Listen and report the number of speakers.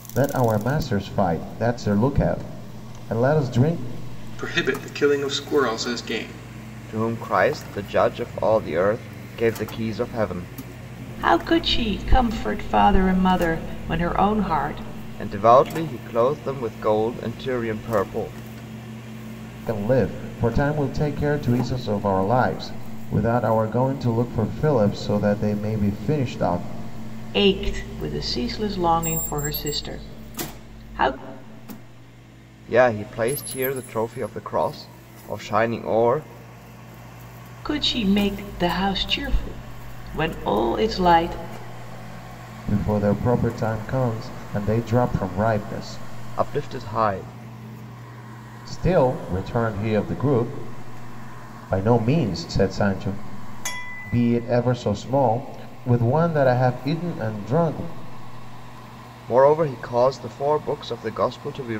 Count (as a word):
four